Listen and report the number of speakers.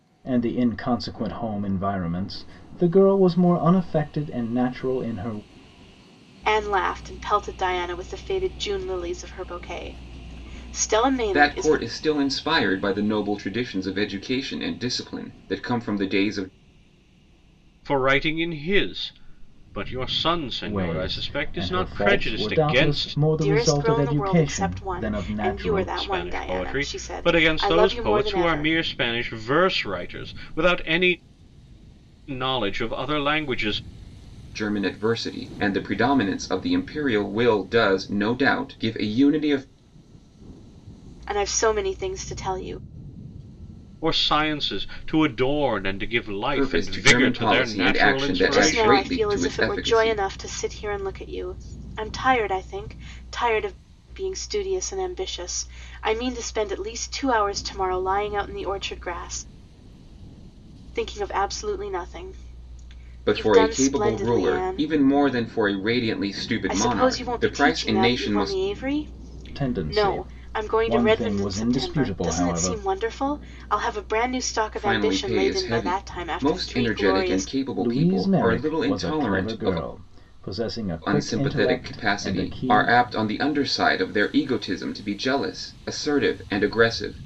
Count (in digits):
4